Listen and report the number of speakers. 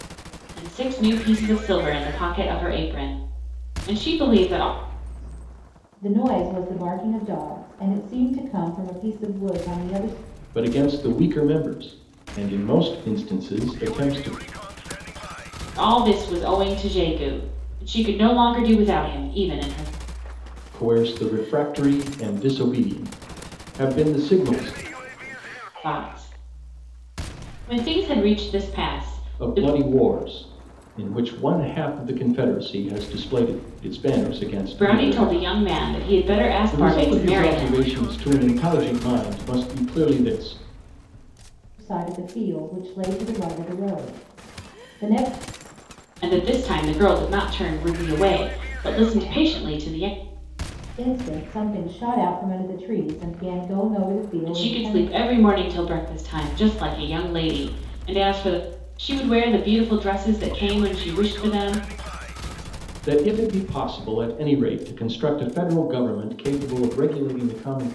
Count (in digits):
3